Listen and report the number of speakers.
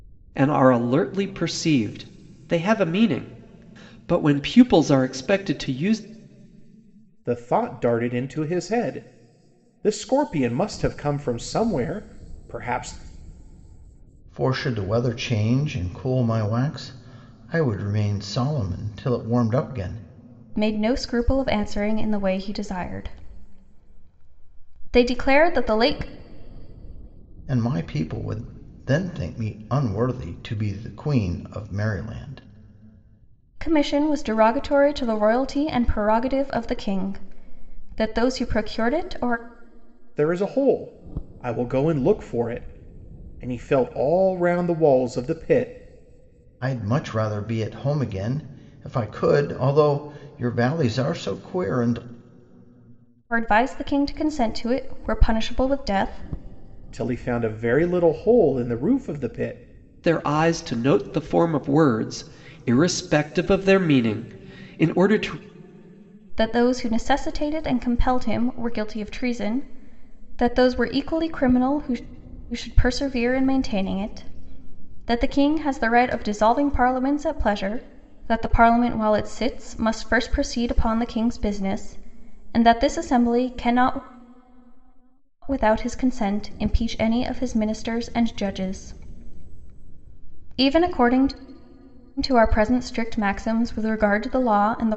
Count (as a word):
four